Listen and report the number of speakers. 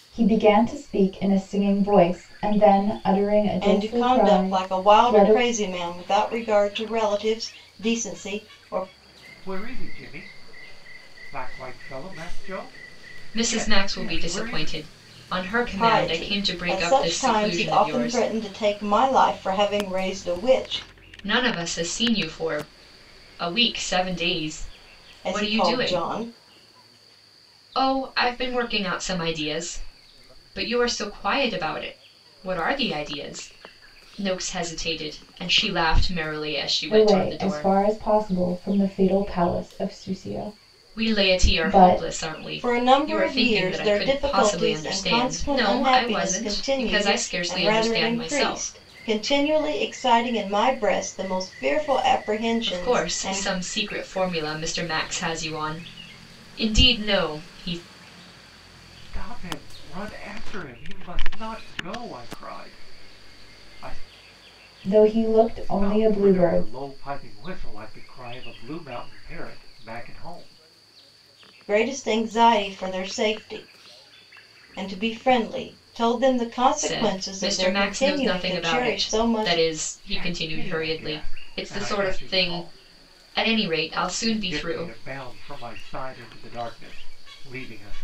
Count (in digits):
4